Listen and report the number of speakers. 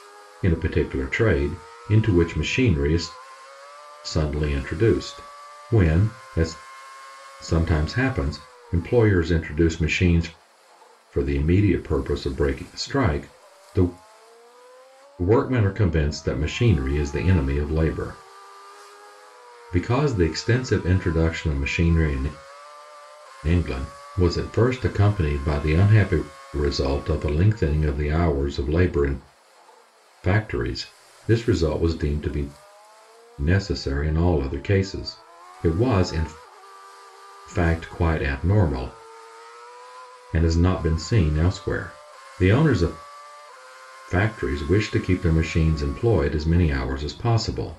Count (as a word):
one